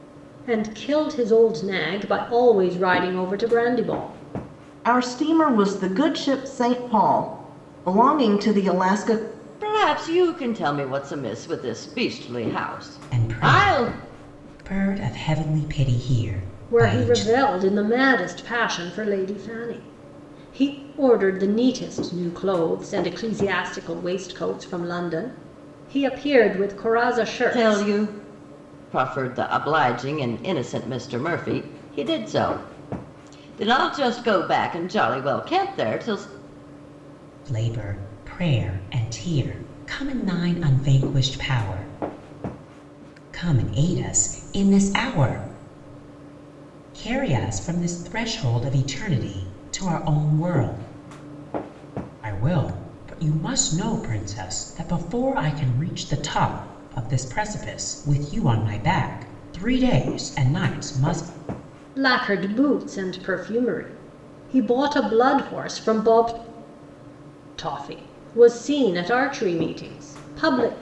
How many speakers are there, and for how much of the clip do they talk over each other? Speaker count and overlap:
four, about 3%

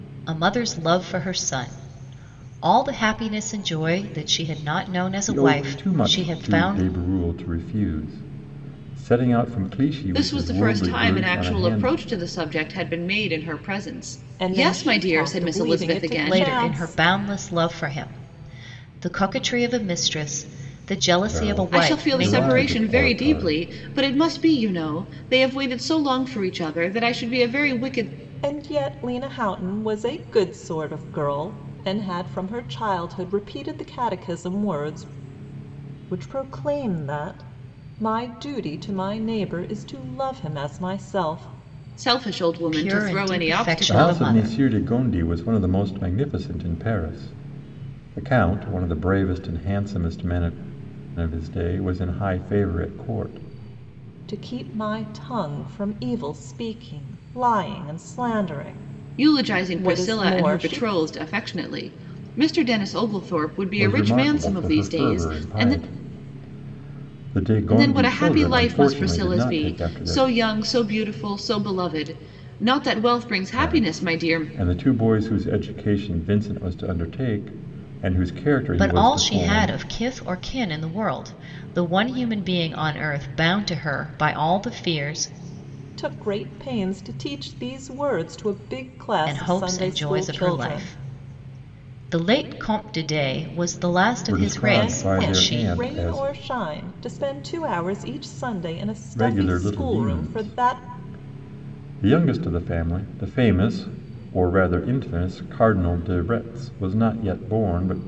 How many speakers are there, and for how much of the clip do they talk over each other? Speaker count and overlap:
four, about 23%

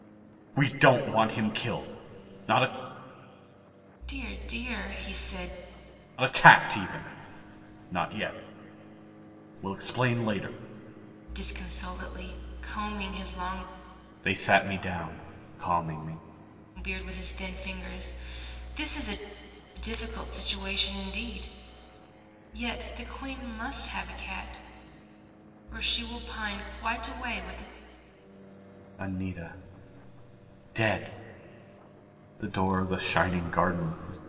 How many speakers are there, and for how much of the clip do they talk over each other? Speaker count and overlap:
two, no overlap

